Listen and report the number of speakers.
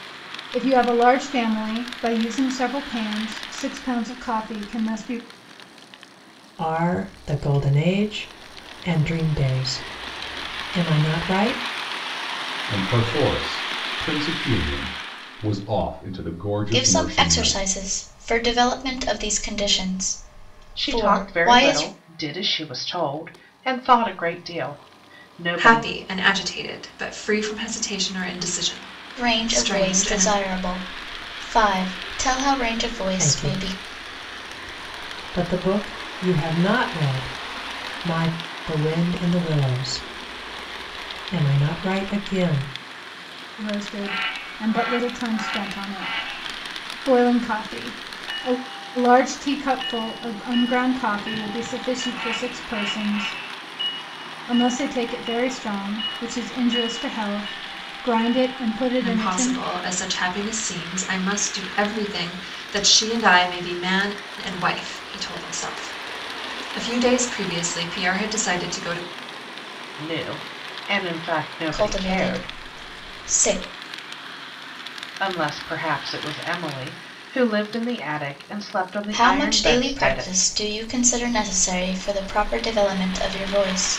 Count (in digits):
6